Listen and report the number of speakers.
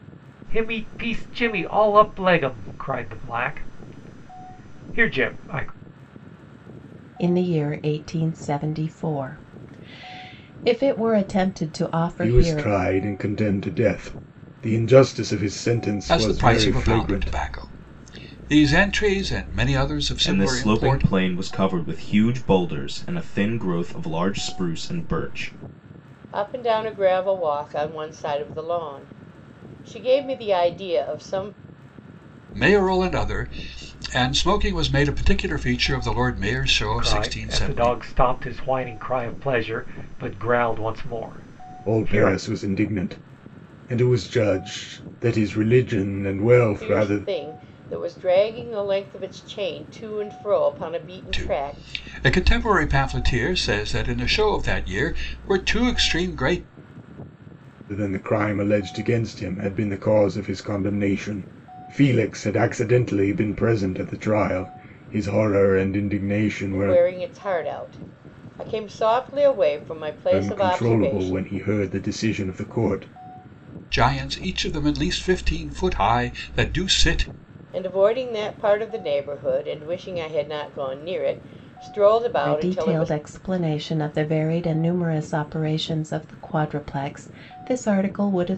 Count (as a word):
six